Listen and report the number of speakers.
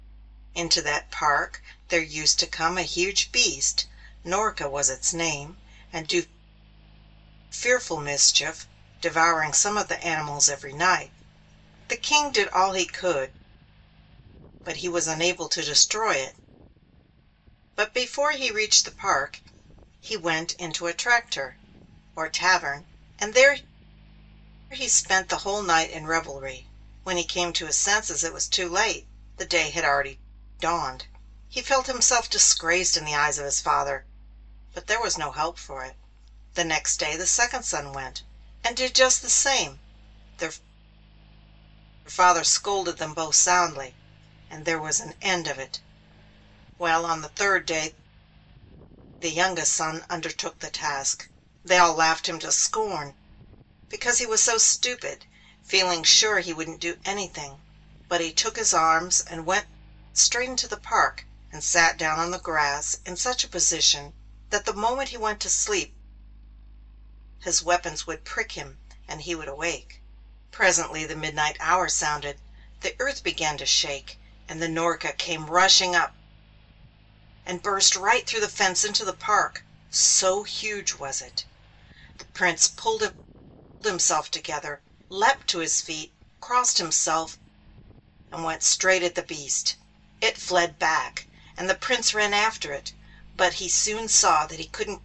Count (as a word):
one